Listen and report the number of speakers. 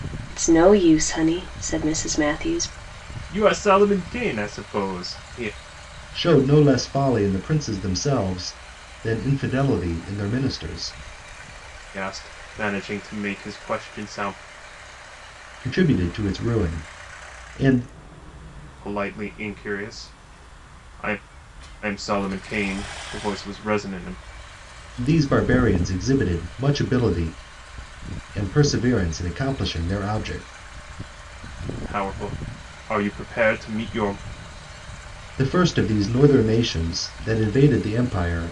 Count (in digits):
3